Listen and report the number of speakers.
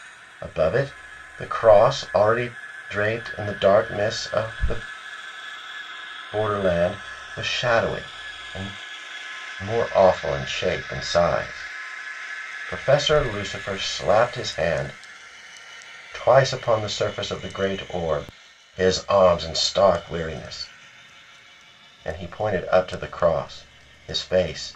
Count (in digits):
1